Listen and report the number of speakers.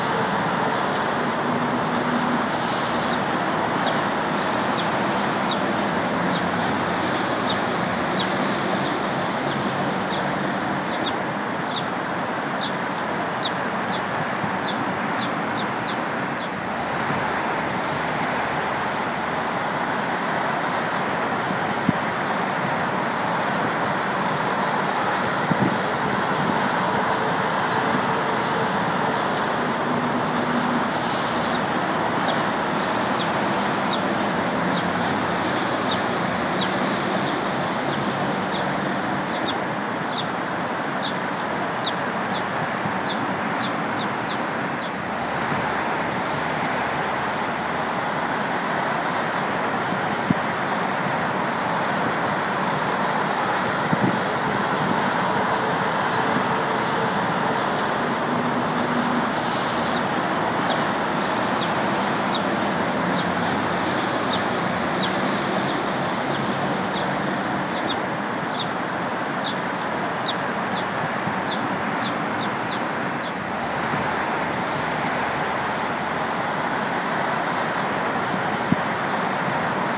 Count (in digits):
0